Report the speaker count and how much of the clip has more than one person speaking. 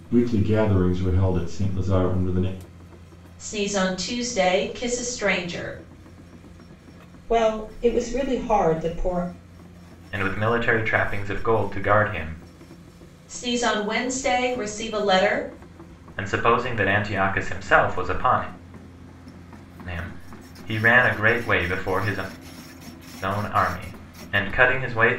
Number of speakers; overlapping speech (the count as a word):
four, no overlap